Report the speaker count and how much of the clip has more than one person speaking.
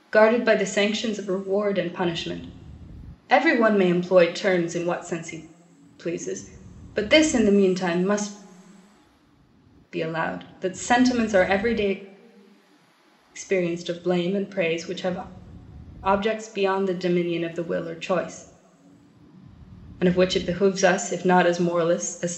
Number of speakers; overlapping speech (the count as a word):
one, no overlap